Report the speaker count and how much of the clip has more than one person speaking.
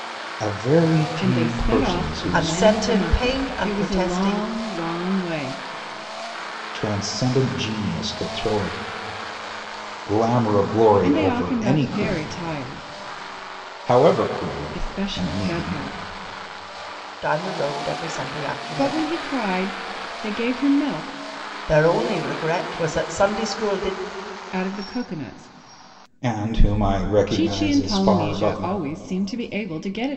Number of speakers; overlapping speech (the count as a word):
three, about 25%